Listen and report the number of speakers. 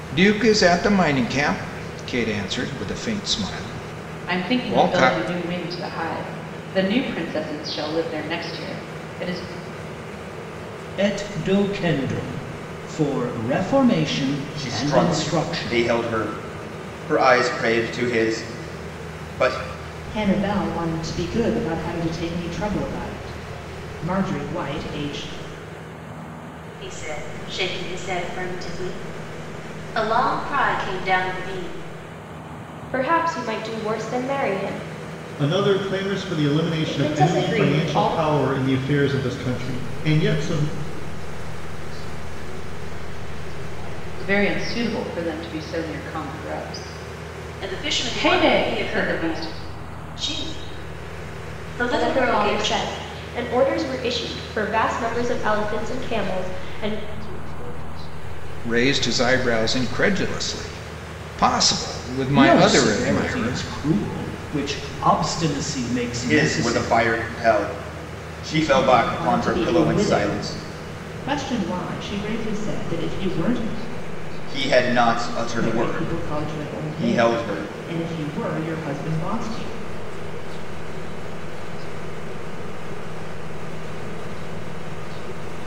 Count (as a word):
nine